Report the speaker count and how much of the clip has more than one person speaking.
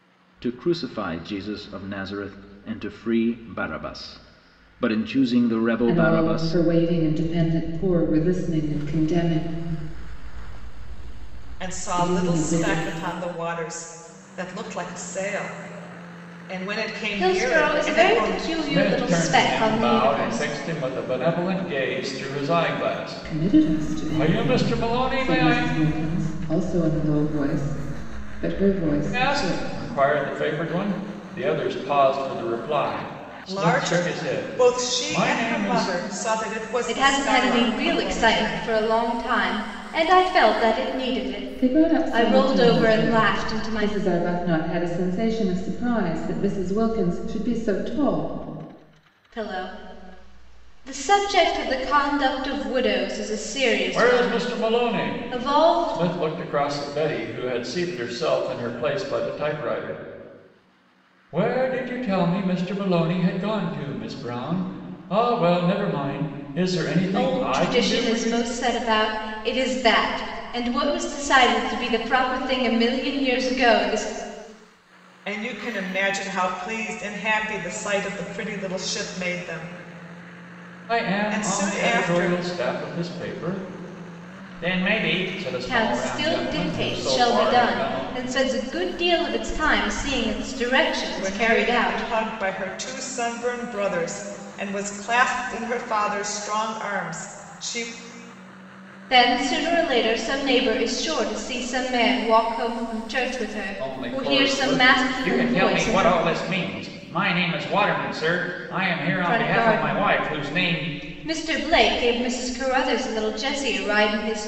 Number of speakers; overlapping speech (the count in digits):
5, about 24%